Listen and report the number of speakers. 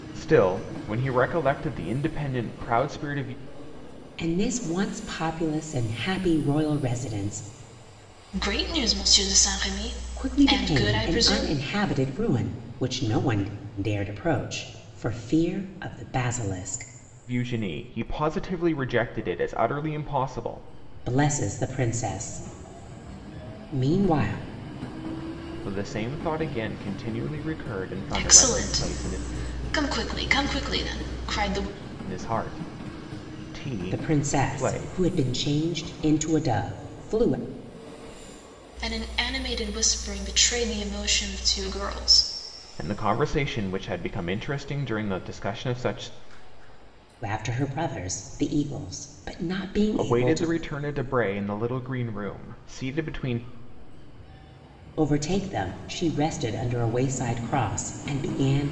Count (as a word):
three